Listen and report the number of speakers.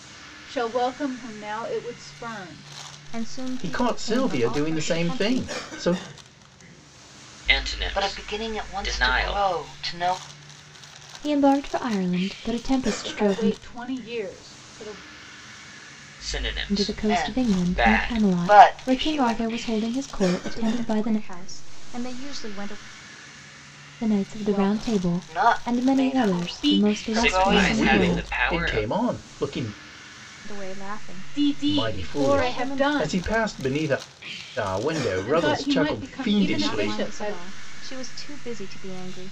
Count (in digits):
6